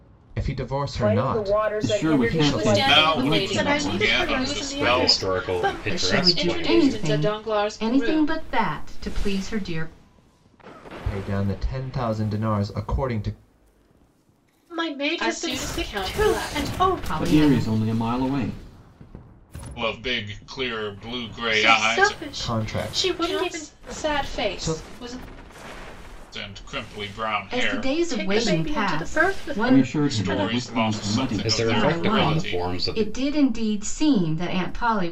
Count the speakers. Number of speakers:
8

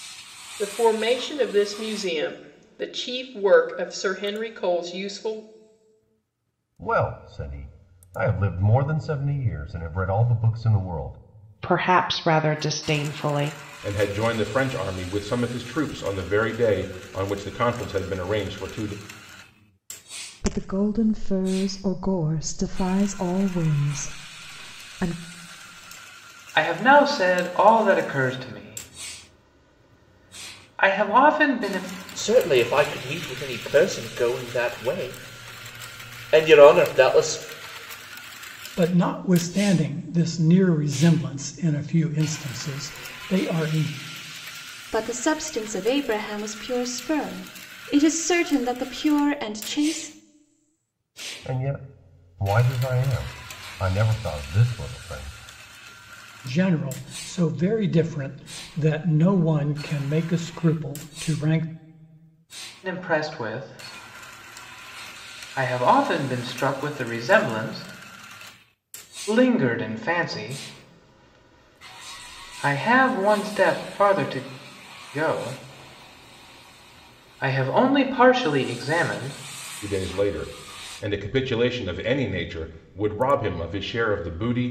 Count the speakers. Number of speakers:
9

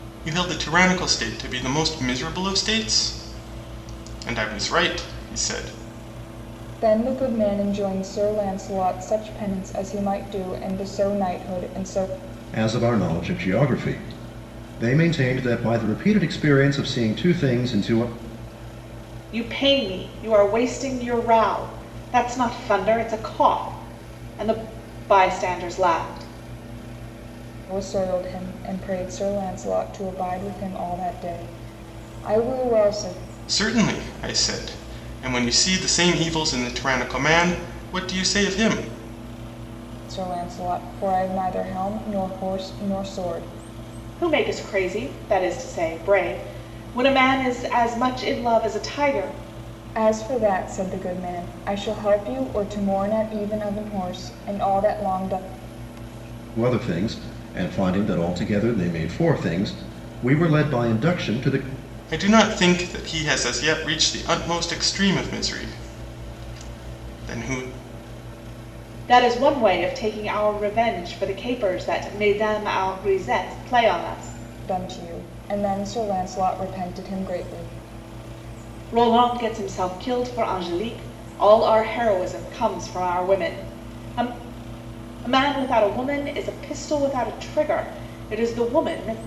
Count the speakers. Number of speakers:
4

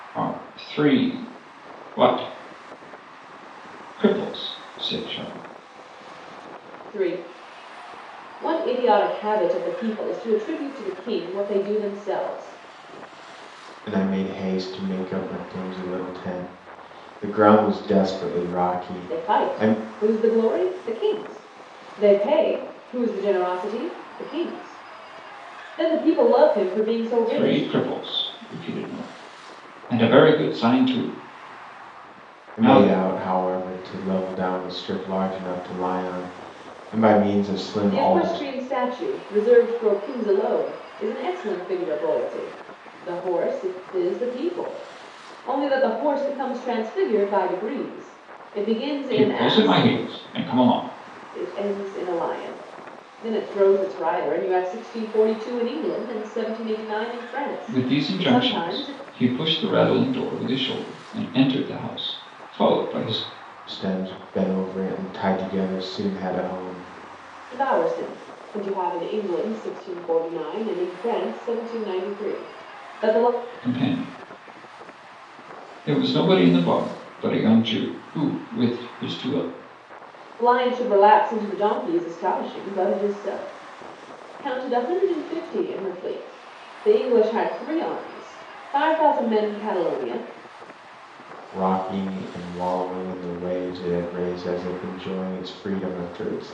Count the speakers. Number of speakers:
3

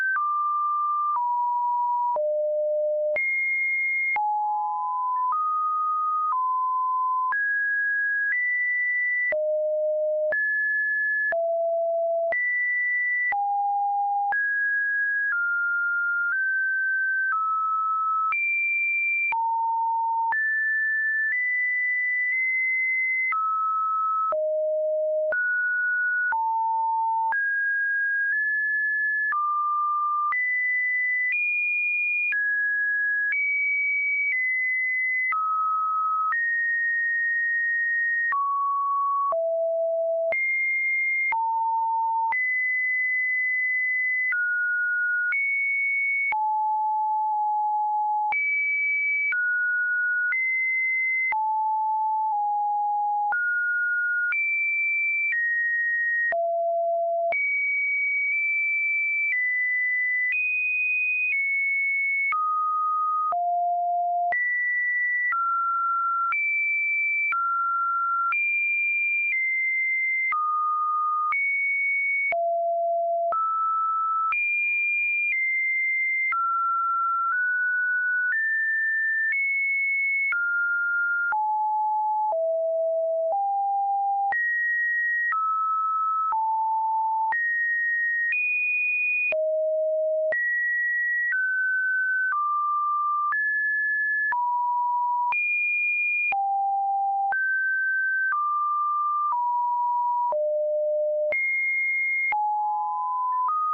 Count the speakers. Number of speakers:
0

